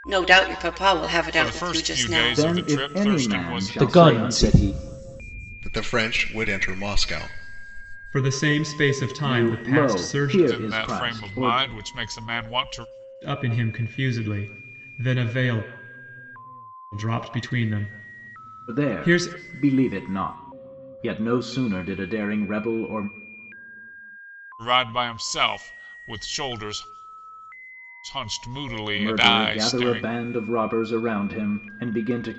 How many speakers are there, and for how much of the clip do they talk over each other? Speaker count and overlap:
six, about 23%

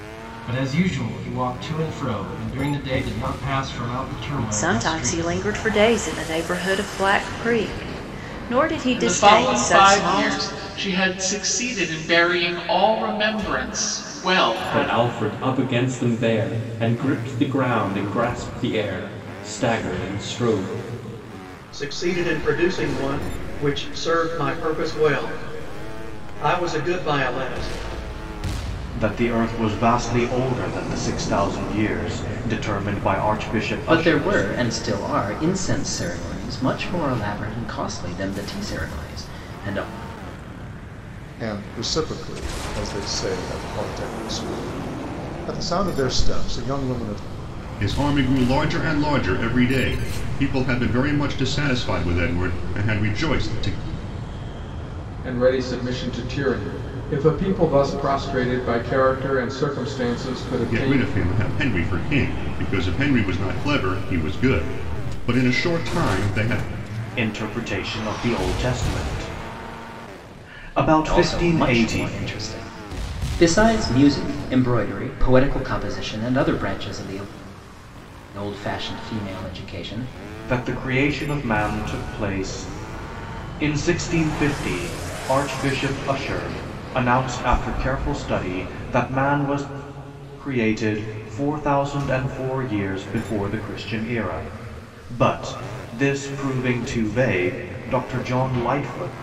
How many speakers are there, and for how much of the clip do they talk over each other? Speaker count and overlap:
ten, about 5%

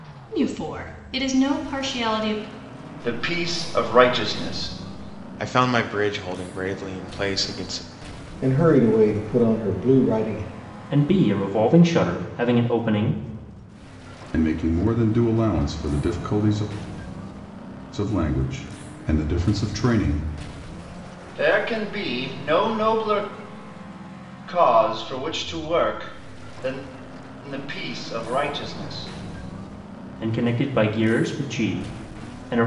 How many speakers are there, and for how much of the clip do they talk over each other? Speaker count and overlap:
six, no overlap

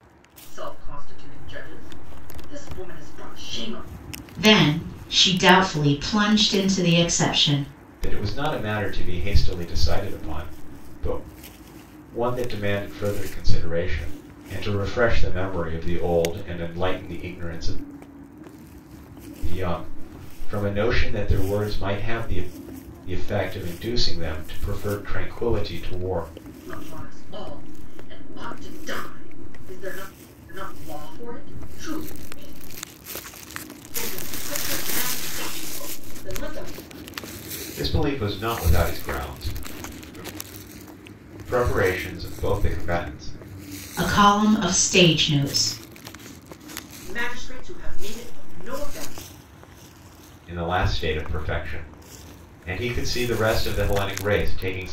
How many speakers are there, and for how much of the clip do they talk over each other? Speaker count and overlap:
three, no overlap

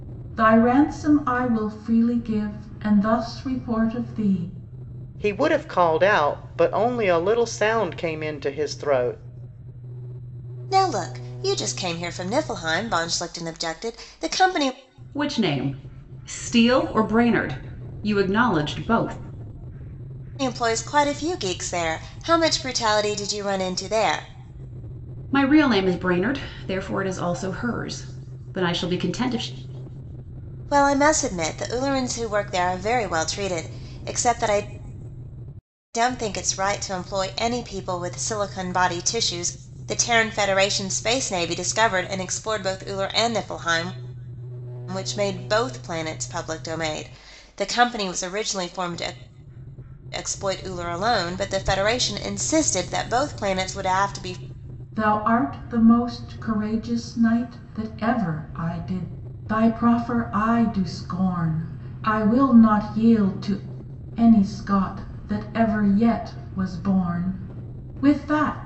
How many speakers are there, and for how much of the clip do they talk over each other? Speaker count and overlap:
four, no overlap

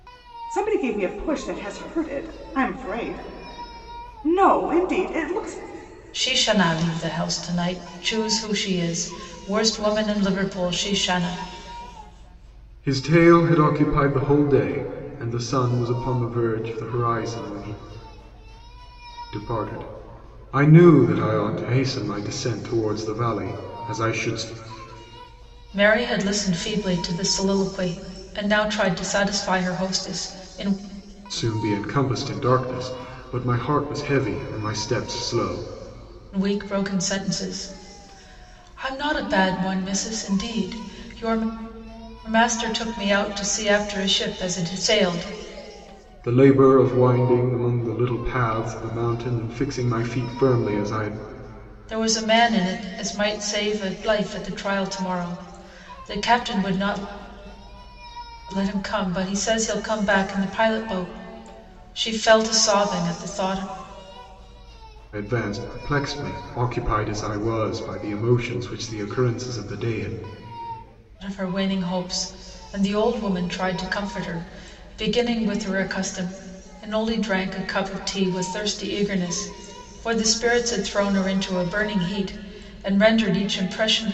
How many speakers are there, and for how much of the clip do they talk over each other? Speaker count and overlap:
three, no overlap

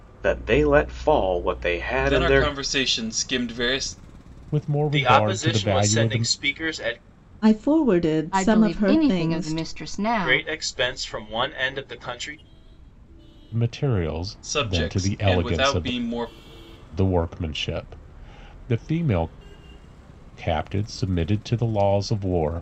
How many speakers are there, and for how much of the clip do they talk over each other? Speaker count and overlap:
six, about 23%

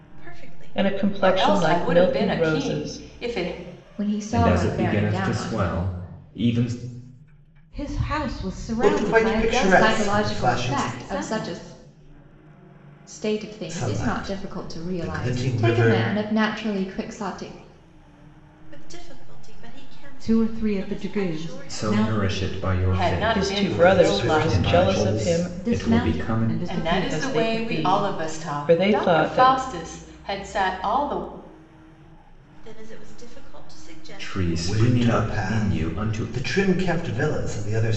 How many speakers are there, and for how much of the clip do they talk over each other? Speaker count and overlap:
seven, about 54%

